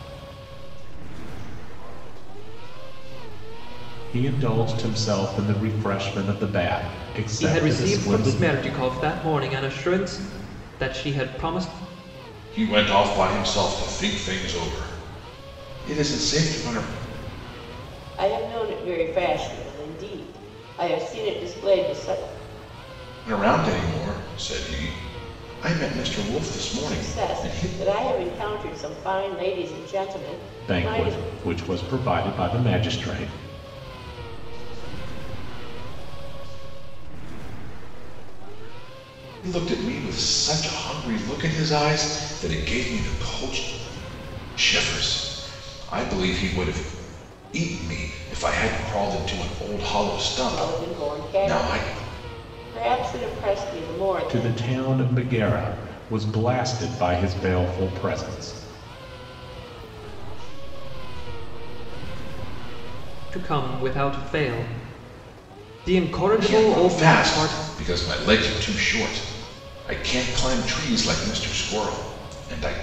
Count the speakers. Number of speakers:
five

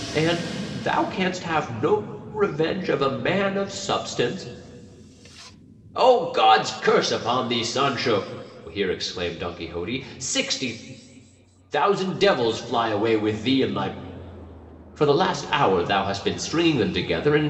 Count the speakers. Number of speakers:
one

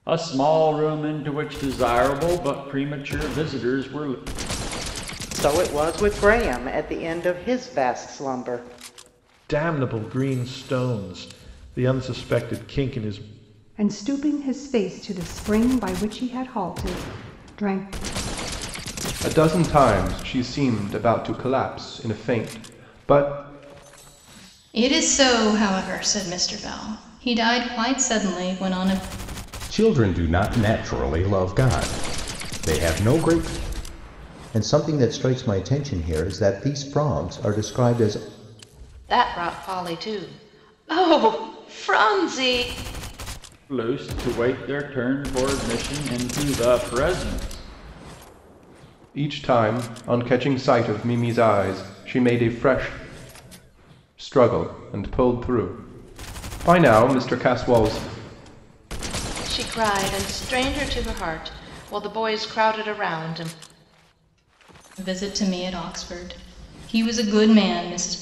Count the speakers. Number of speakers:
nine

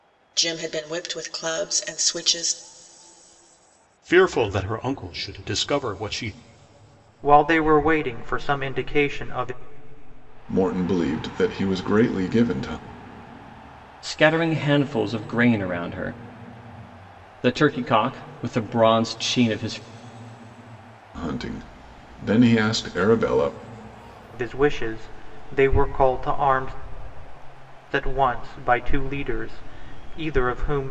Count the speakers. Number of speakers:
five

